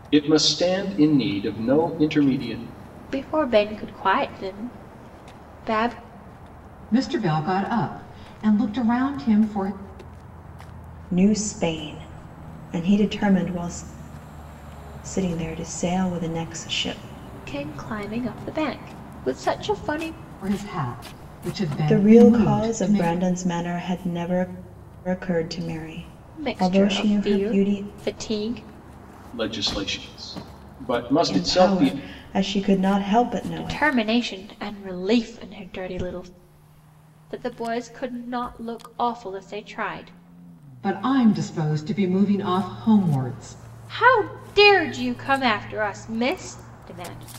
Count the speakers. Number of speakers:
4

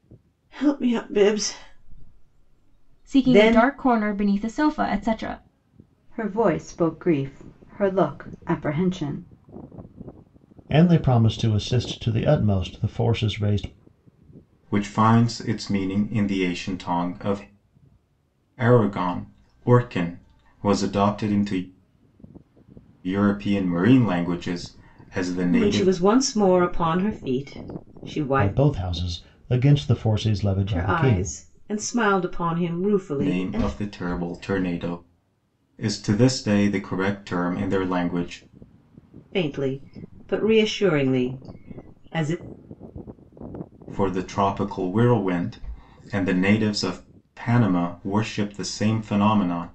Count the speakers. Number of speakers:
5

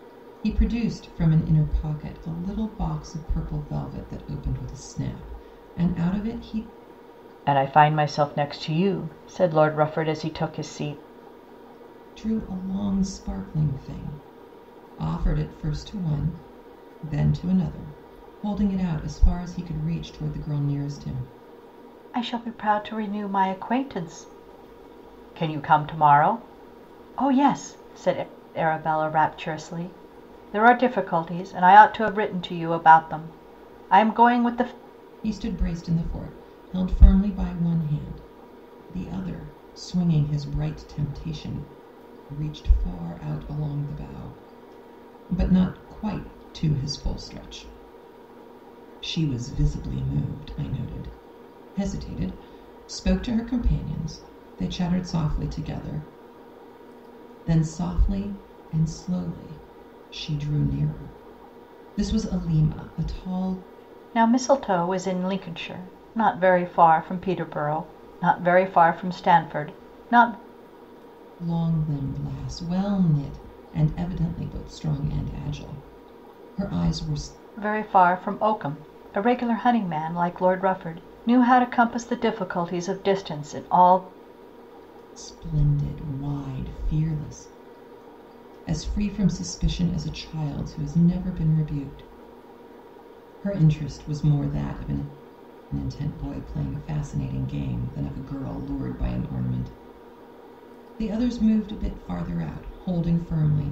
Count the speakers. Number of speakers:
2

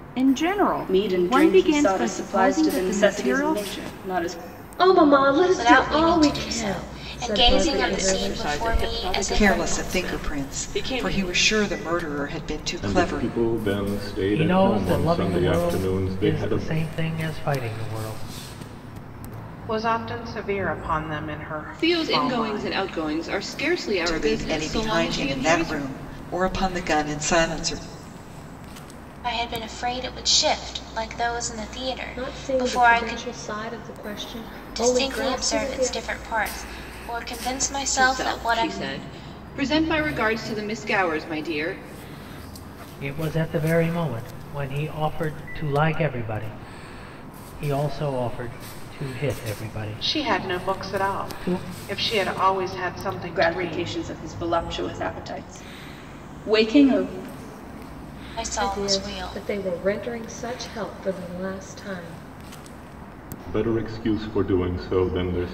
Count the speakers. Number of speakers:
10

